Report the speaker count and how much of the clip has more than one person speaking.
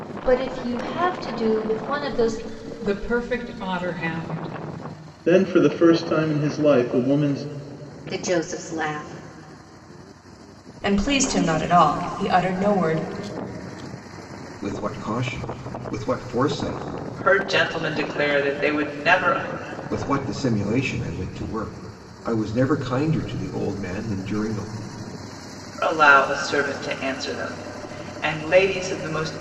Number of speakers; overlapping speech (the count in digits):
7, no overlap